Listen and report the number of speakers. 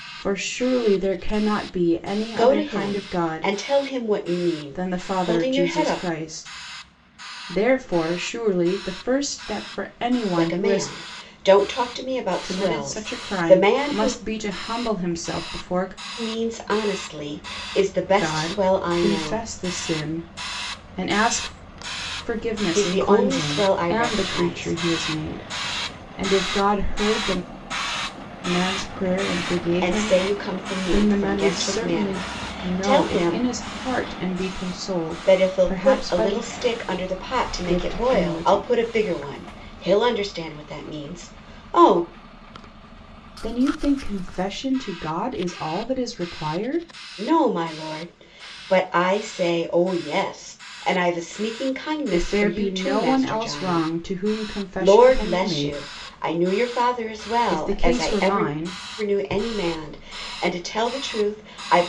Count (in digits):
2